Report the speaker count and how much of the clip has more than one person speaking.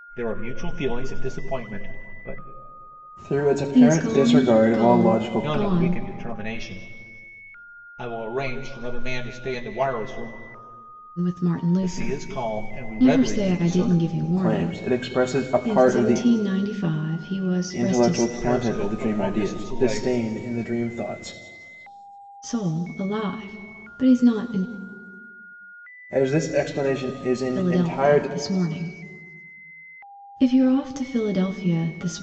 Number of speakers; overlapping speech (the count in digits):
3, about 30%